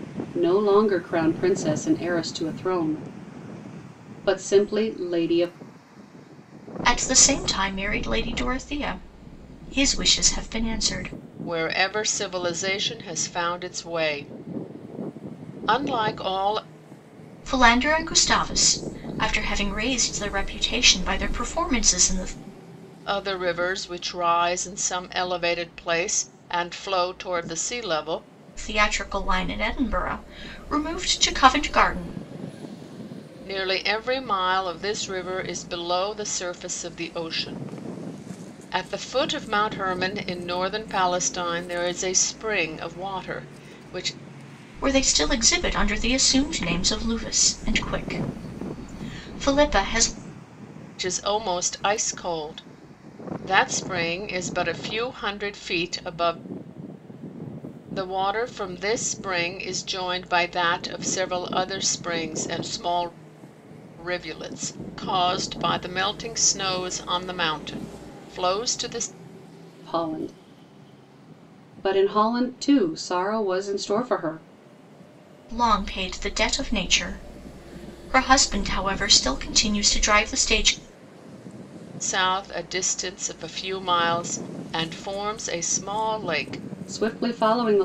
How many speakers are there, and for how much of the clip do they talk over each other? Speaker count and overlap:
three, no overlap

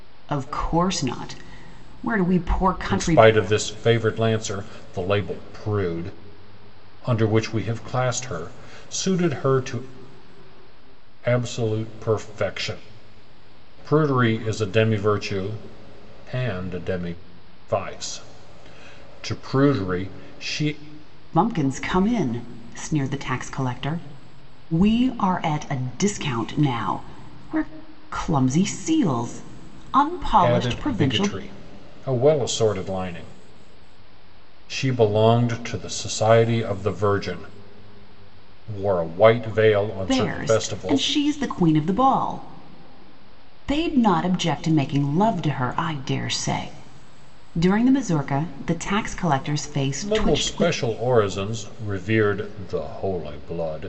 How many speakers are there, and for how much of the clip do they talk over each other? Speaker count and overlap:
two, about 6%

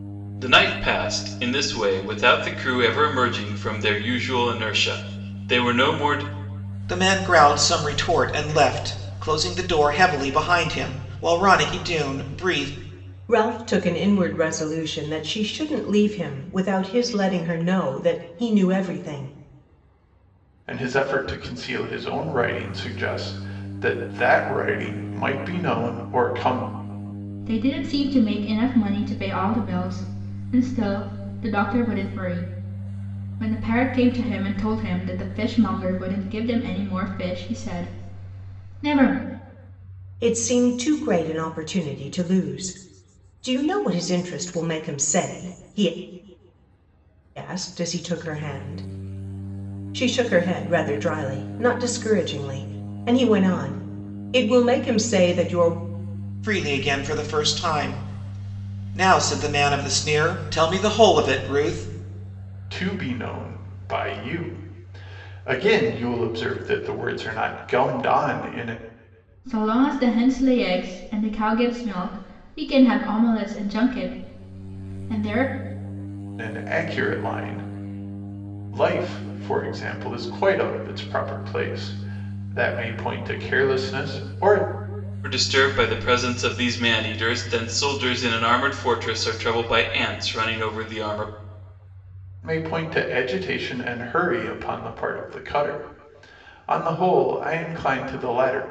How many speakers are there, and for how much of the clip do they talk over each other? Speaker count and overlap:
five, no overlap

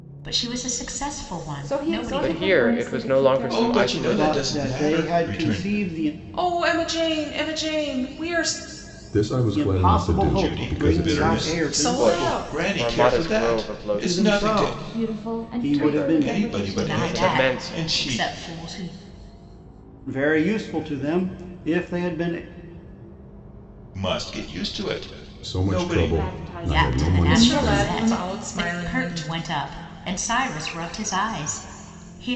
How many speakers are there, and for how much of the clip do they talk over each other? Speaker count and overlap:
seven, about 51%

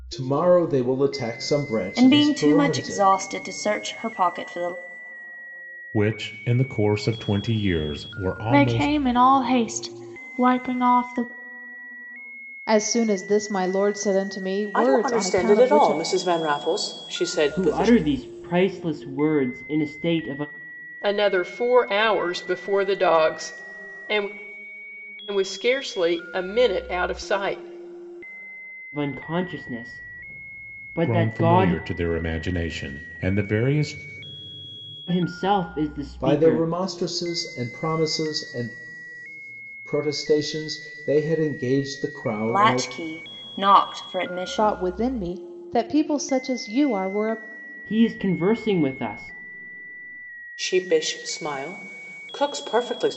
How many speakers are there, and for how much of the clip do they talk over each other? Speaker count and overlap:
eight, about 11%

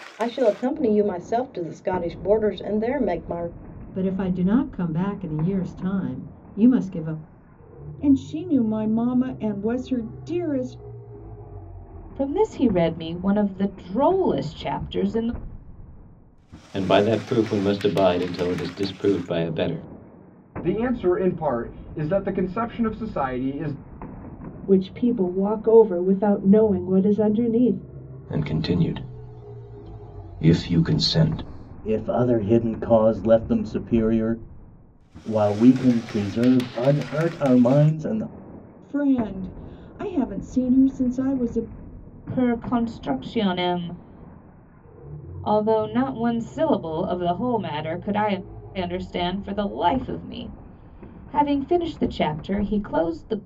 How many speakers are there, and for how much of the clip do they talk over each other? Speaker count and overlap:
nine, no overlap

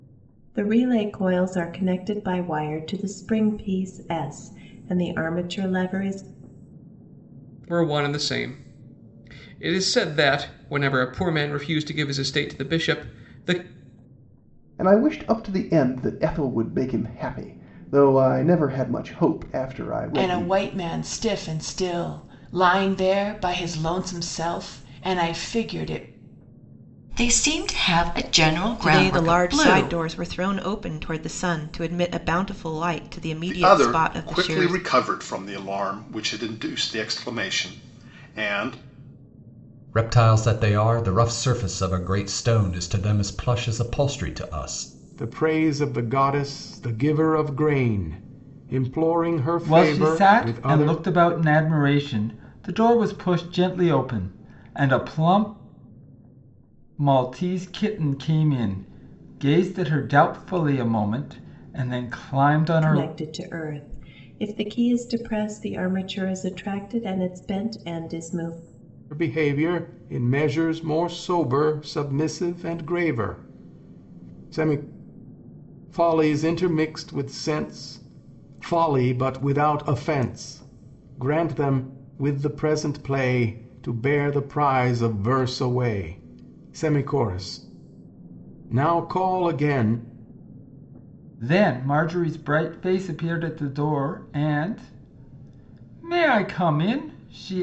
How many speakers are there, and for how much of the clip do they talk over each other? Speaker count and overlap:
ten, about 5%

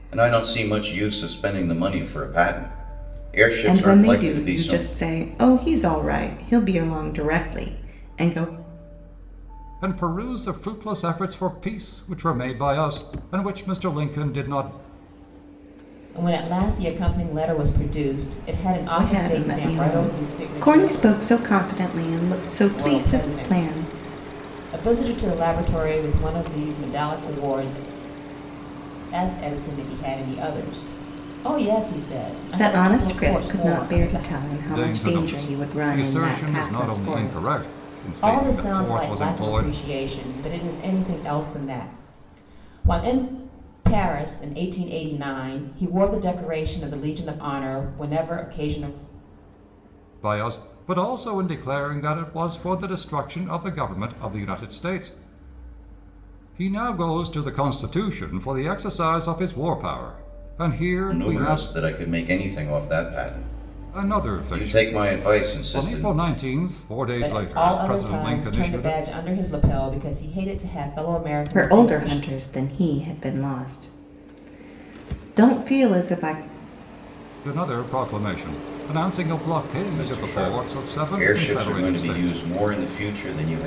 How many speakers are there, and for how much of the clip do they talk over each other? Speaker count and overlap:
four, about 22%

